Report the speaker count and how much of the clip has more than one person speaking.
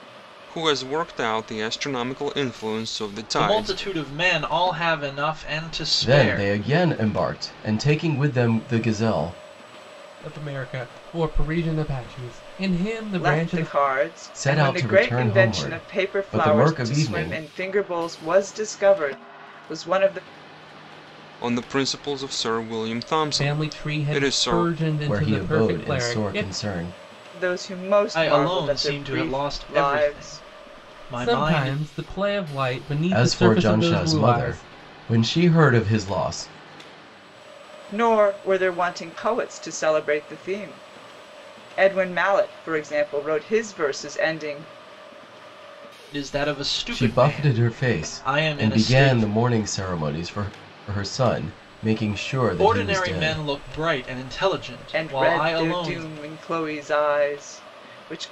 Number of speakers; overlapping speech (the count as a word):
five, about 28%